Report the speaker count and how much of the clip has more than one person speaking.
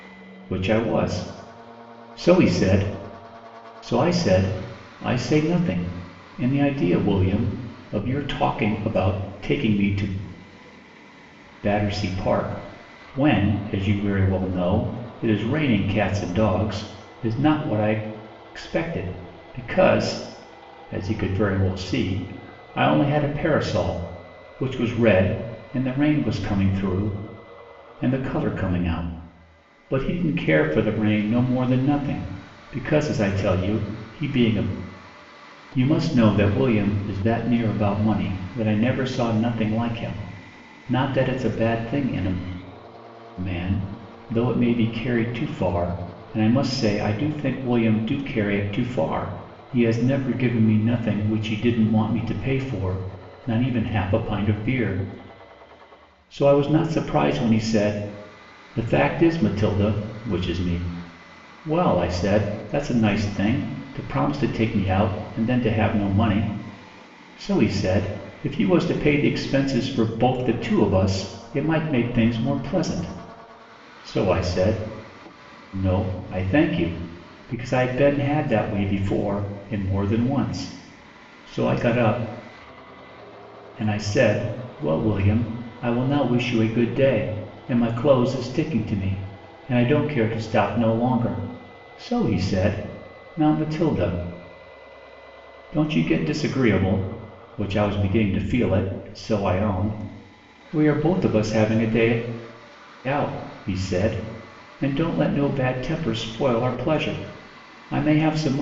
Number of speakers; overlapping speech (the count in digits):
1, no overlap